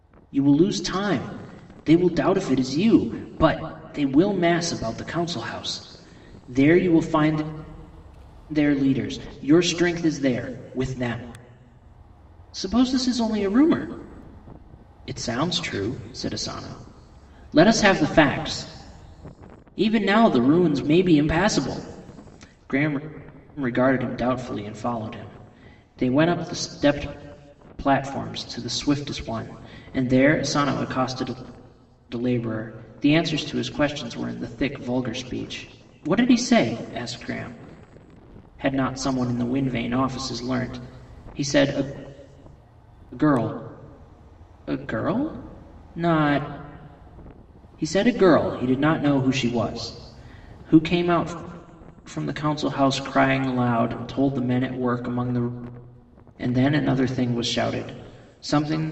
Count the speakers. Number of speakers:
1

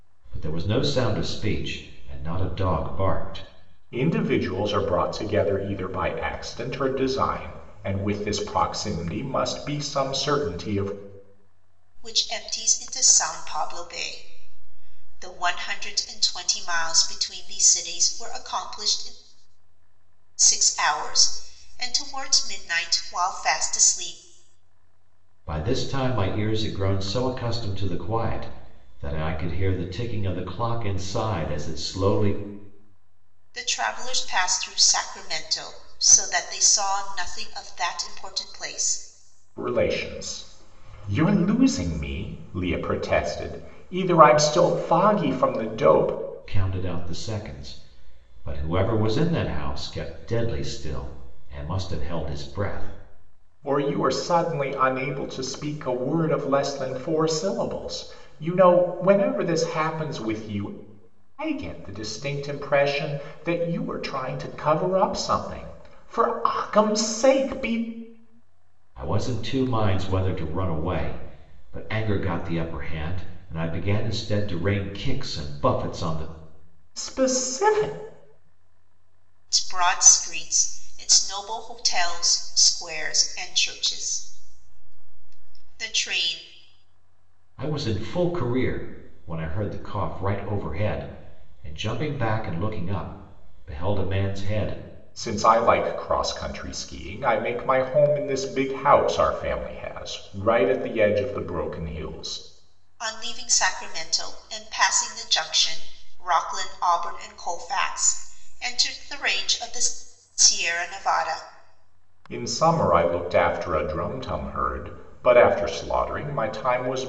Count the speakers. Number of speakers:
3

